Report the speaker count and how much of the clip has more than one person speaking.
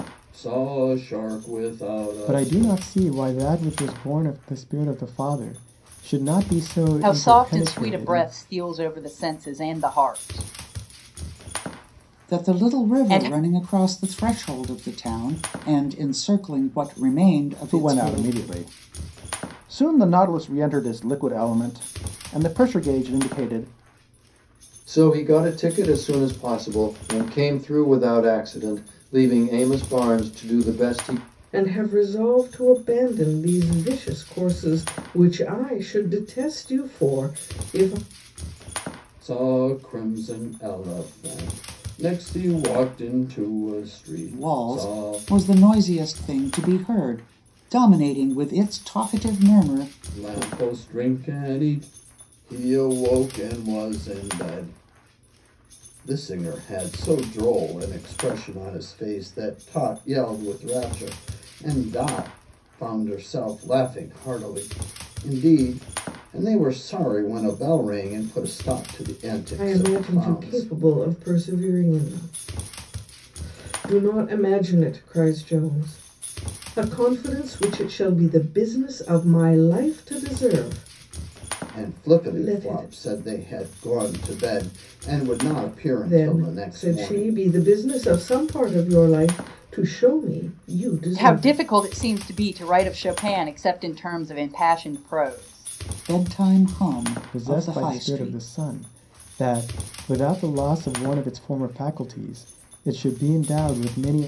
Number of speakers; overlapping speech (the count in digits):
7, about 10%